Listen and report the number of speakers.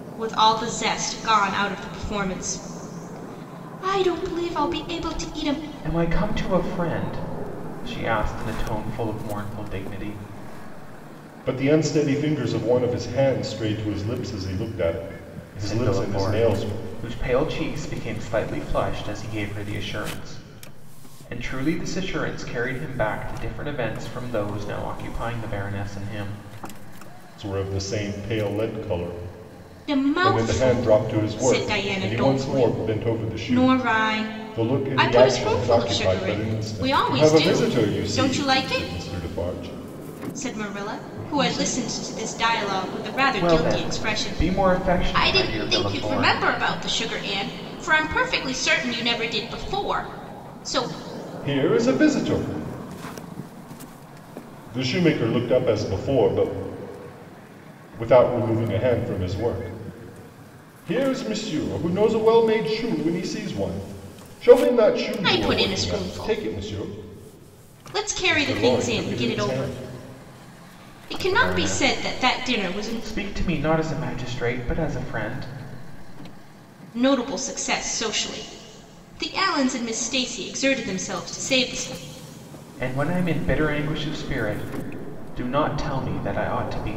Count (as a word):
three